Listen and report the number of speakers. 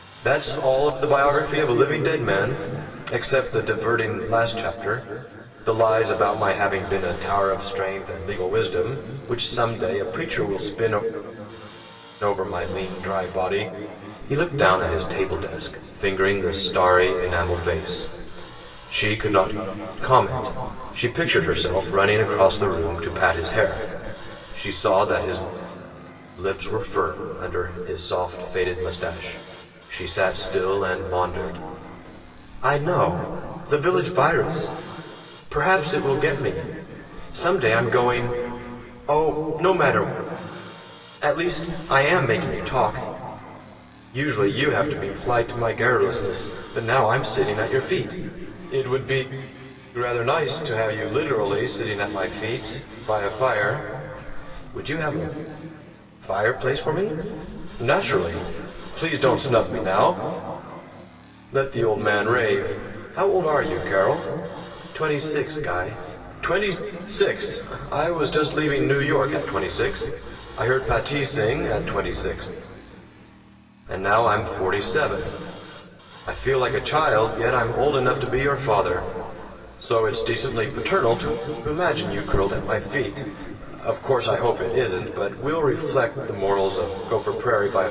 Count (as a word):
one